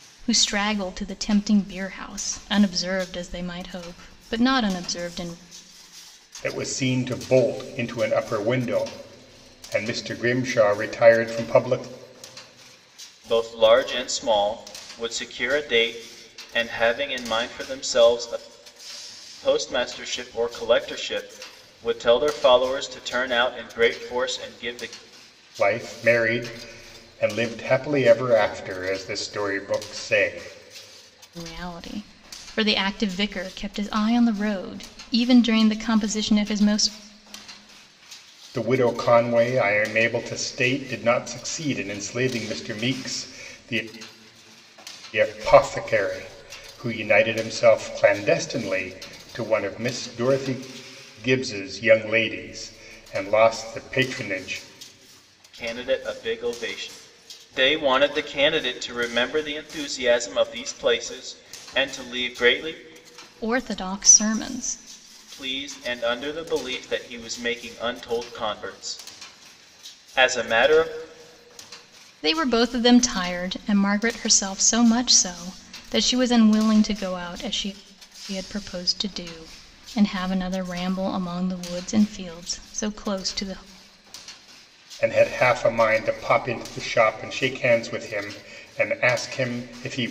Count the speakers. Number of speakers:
three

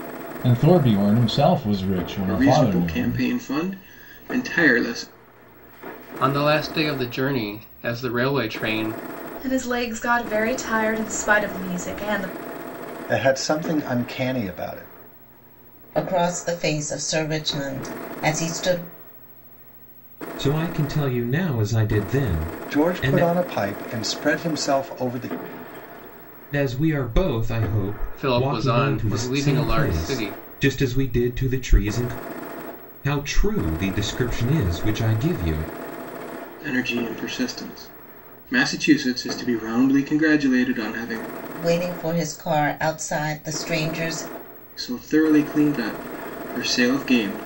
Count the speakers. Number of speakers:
seven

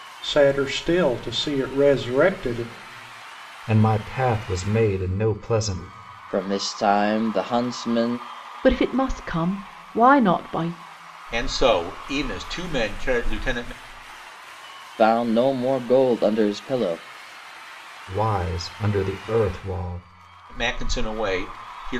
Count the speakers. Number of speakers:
five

